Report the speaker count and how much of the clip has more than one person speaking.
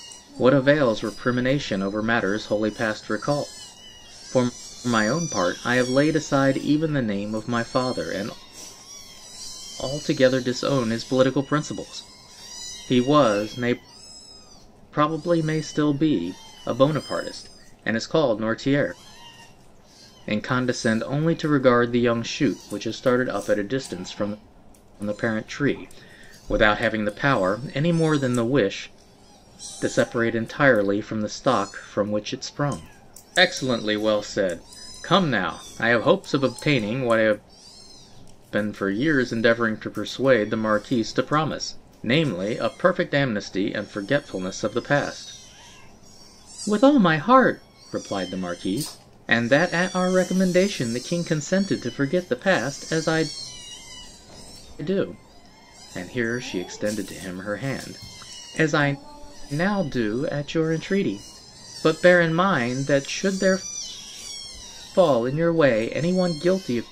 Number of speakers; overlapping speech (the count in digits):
1, no overlap